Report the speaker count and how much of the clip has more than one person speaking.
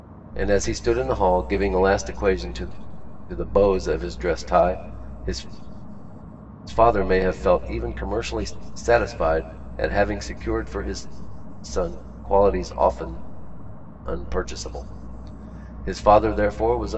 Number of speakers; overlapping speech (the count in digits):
1, no overlap